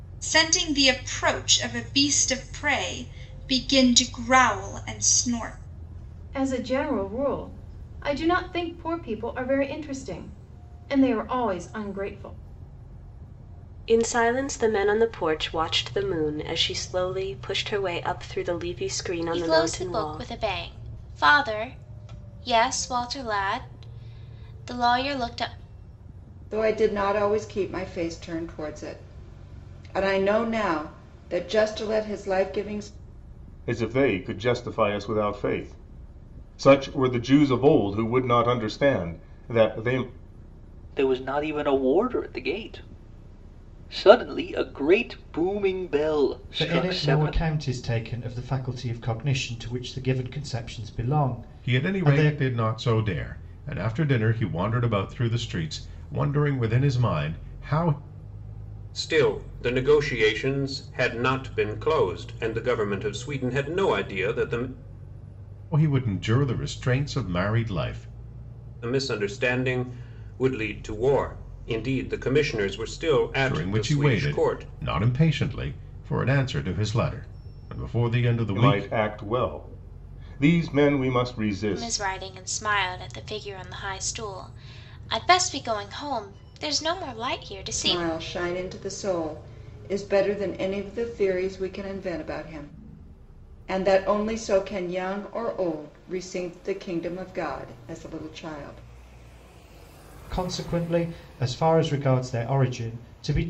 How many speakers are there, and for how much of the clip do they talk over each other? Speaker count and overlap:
ten, about 5%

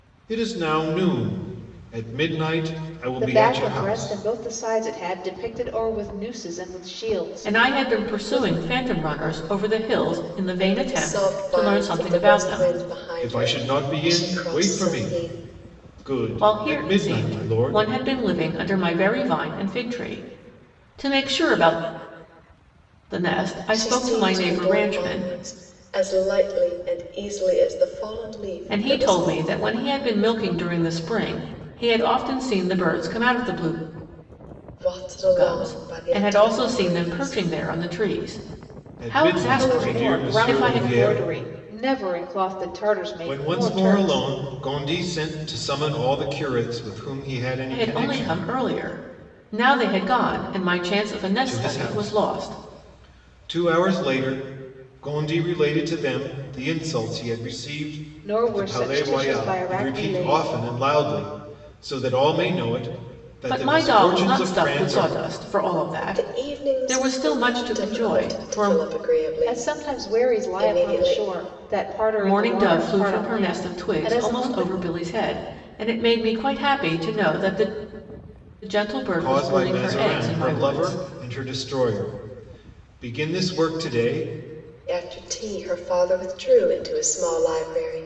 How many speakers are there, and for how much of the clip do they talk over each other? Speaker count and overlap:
four, about 35%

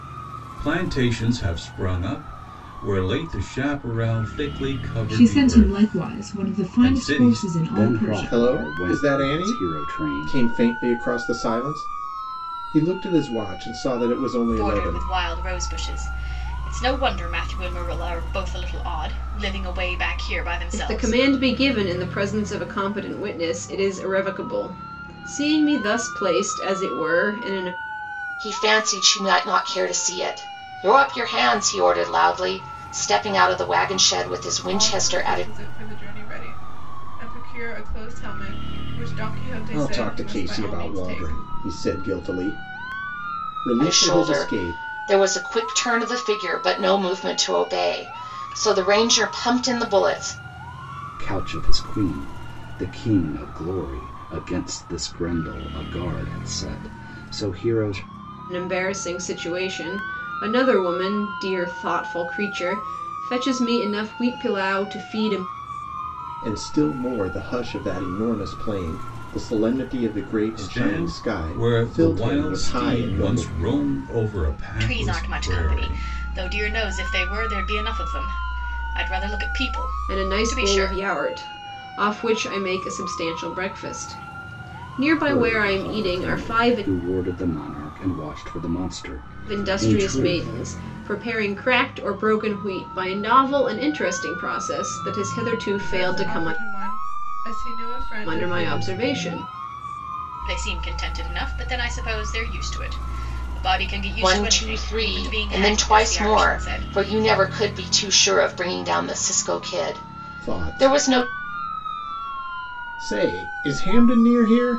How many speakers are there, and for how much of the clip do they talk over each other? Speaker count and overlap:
eight, about 20%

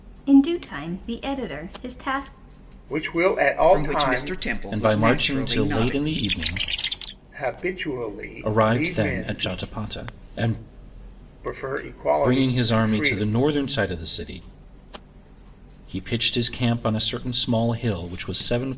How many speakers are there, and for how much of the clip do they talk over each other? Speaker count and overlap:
four, about 24%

